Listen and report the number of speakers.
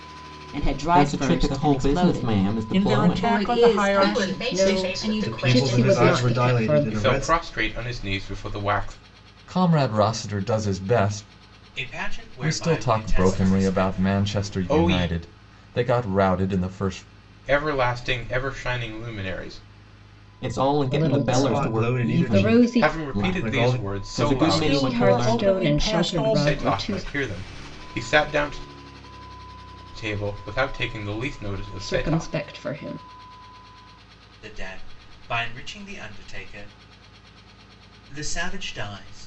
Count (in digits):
10